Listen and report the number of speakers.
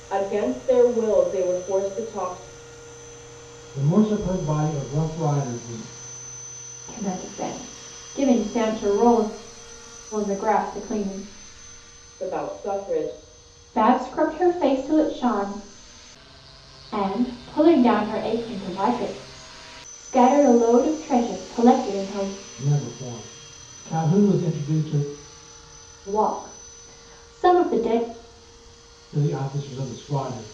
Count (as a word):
three